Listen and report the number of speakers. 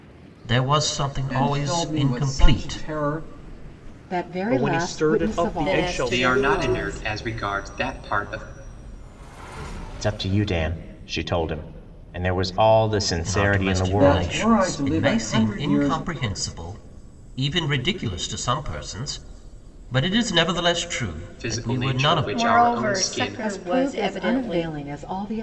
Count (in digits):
7